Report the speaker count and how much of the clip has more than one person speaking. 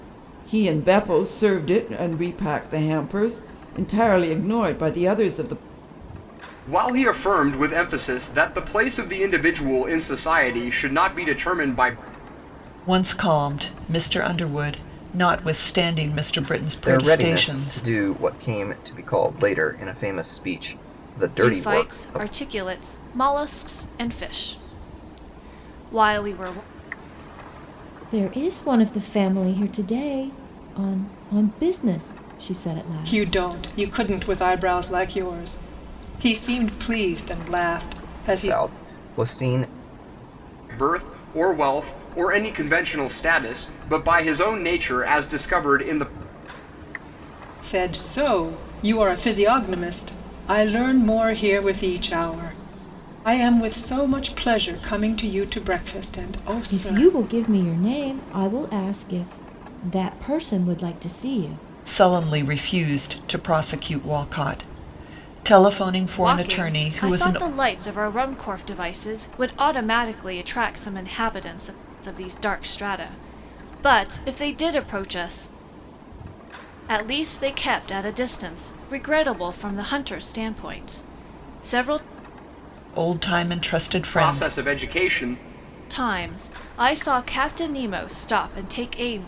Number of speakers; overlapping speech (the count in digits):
7, about 6%